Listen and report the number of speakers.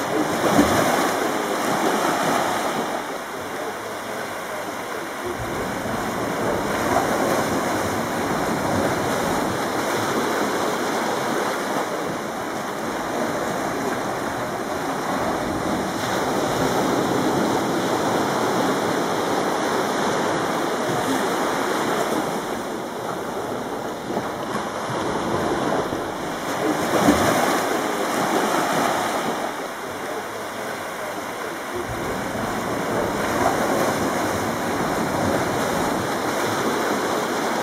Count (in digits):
0